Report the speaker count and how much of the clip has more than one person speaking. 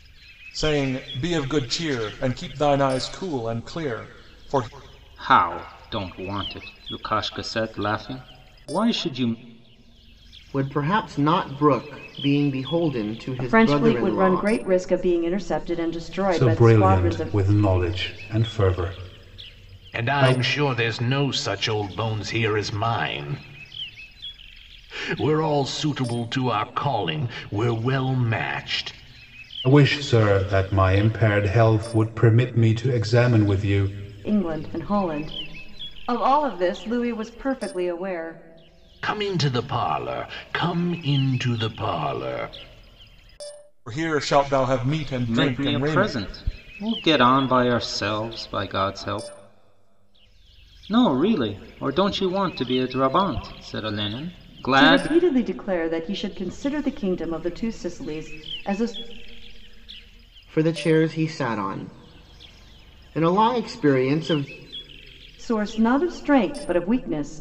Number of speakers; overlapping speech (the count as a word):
six, about 6%